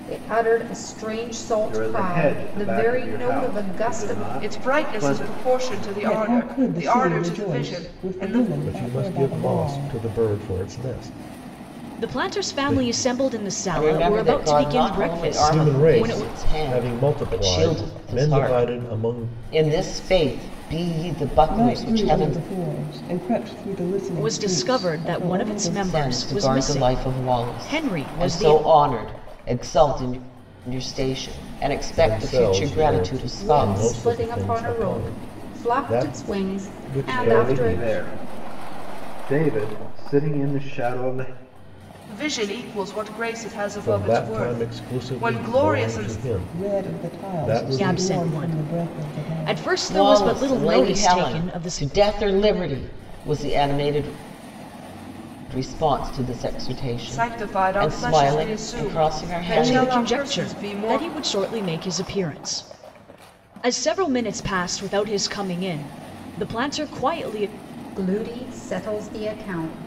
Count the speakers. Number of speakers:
7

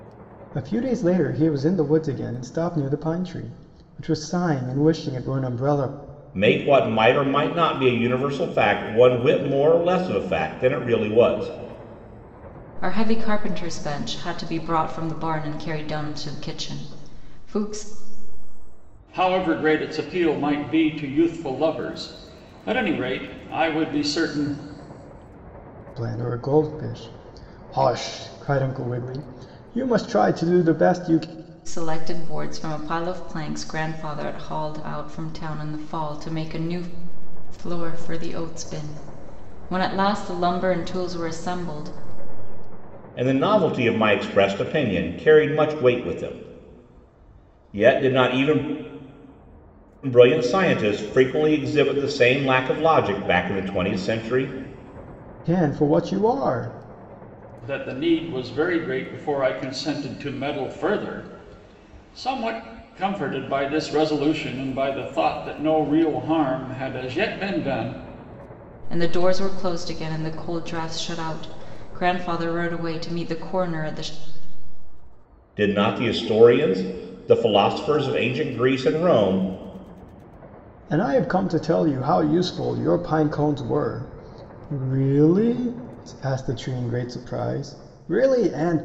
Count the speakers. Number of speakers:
4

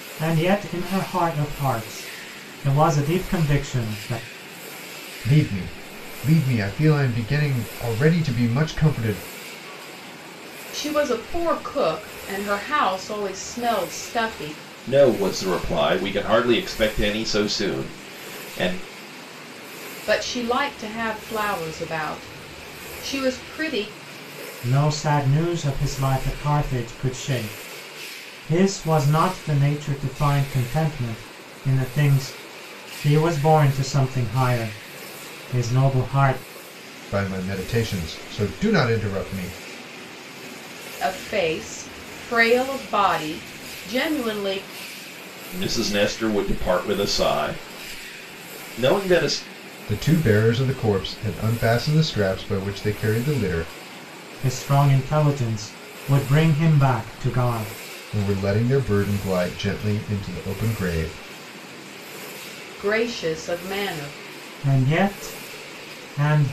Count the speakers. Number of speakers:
4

